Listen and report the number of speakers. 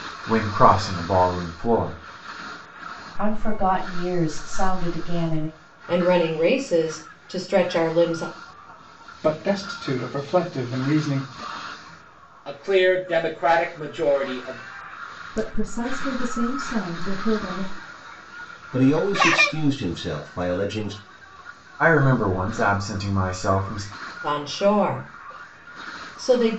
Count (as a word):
seven